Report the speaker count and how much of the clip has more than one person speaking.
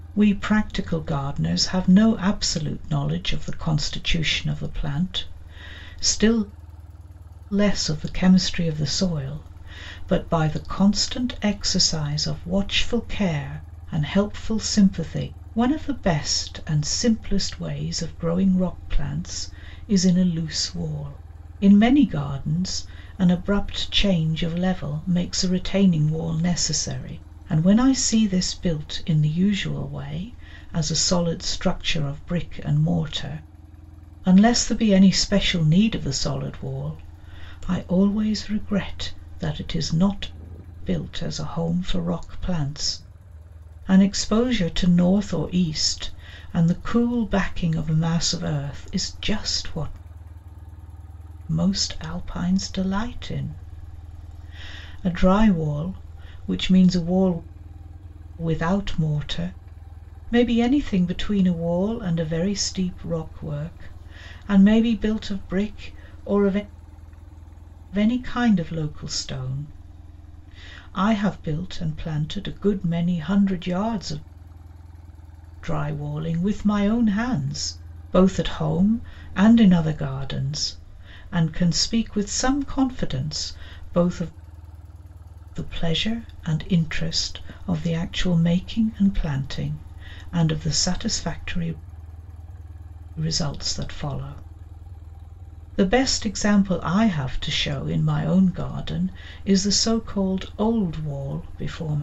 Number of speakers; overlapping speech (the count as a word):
one, no overlap